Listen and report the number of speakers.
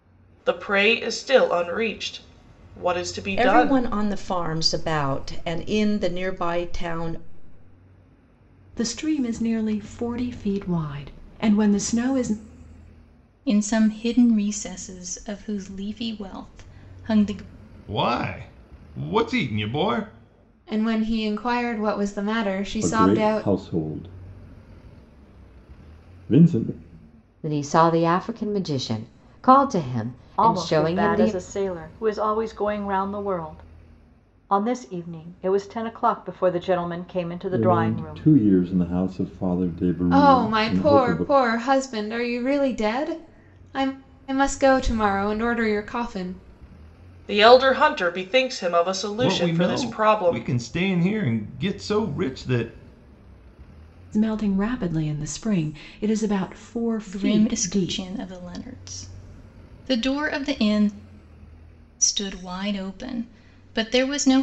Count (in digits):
9